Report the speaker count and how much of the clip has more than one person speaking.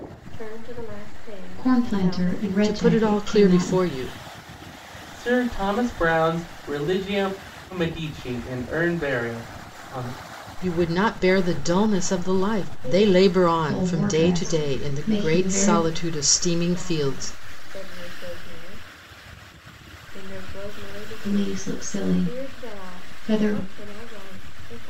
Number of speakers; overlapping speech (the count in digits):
4, about 41%